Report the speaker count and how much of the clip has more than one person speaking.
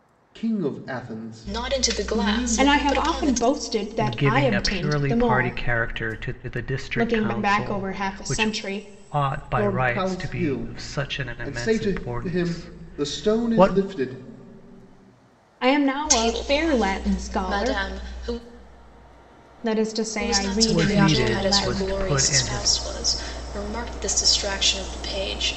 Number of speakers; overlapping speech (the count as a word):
four, about 58%